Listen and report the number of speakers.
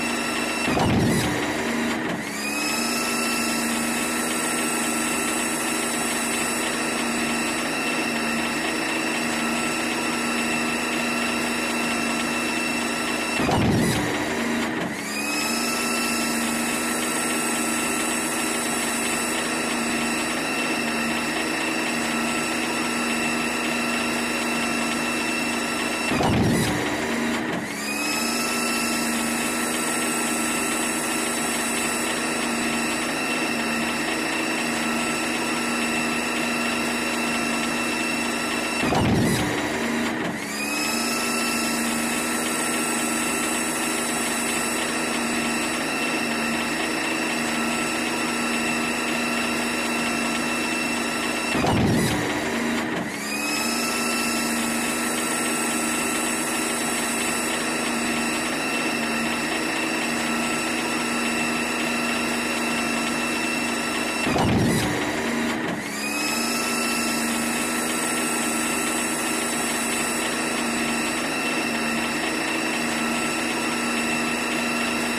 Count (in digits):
0